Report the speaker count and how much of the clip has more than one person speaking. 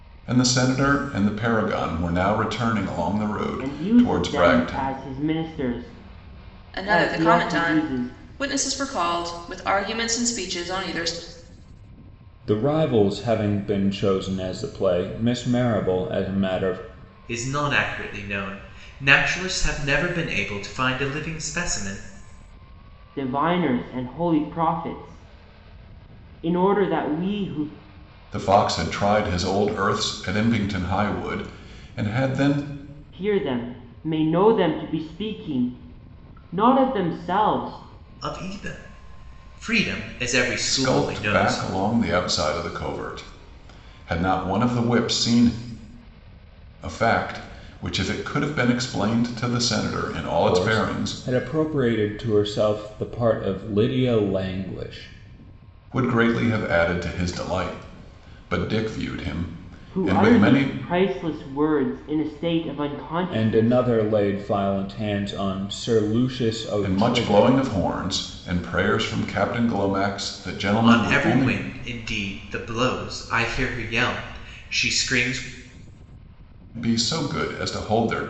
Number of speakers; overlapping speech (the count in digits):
5, about 10%